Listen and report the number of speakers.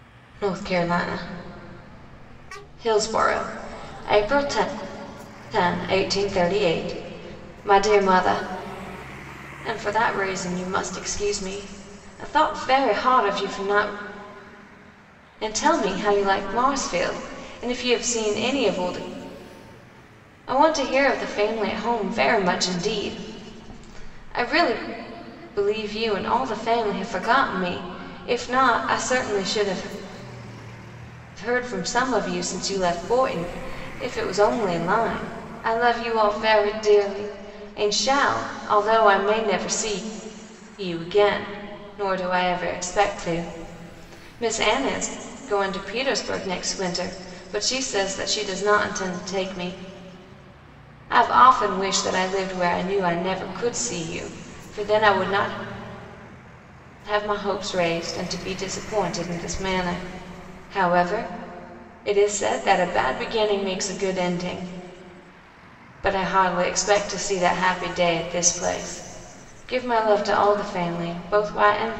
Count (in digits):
1